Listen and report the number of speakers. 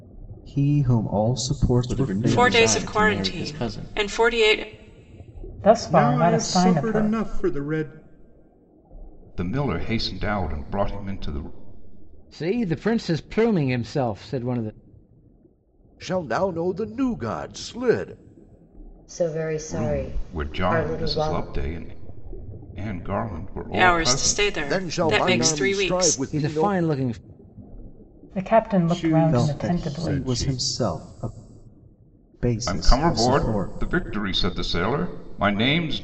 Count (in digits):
9